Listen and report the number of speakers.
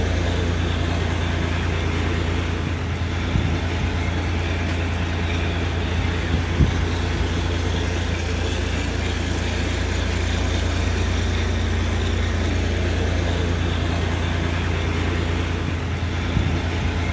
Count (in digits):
0